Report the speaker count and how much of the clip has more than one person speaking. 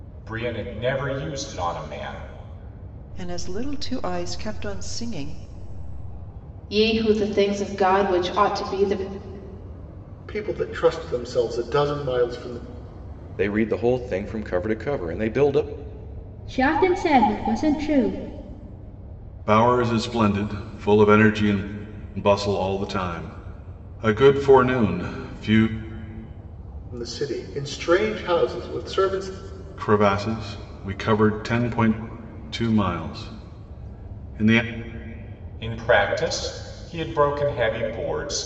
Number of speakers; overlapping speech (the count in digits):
7, no overlap